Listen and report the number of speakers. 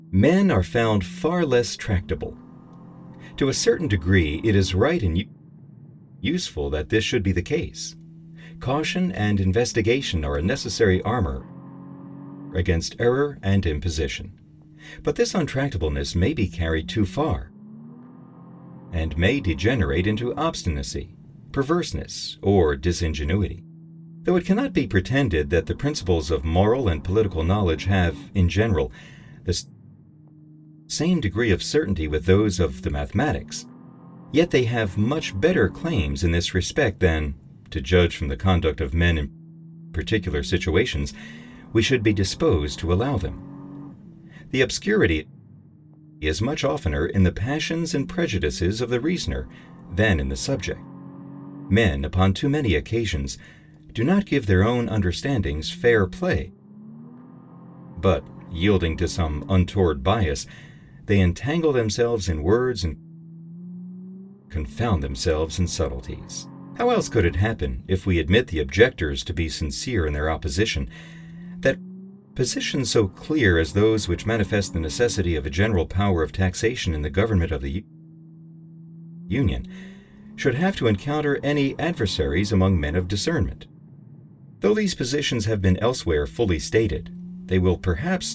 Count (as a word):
one